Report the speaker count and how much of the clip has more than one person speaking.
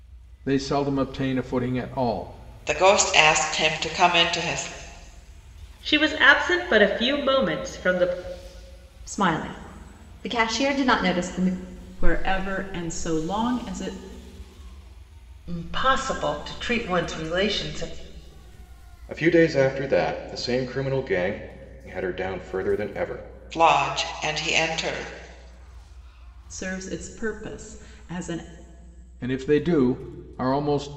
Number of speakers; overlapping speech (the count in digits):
7, no overlap